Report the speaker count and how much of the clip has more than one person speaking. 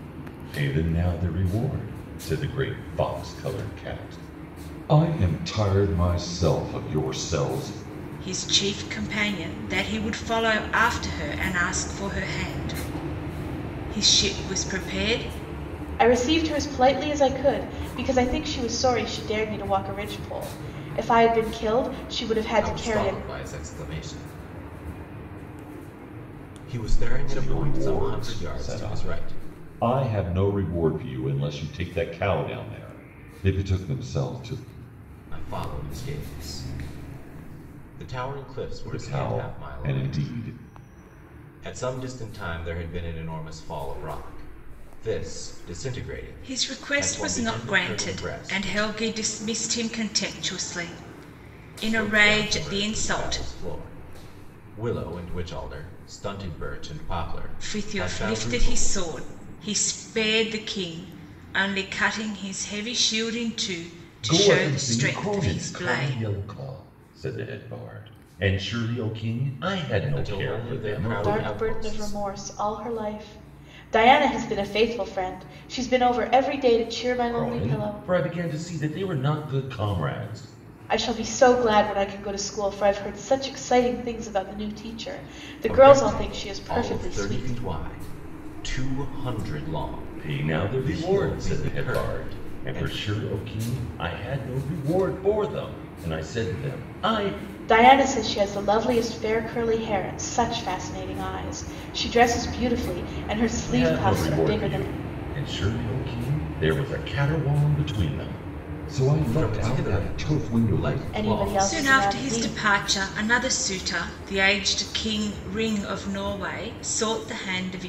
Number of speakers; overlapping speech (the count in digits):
4, about 20%